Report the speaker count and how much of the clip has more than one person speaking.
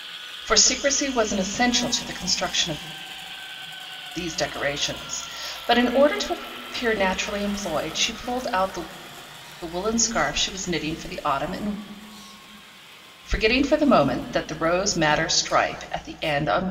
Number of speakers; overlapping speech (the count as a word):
one, no overlap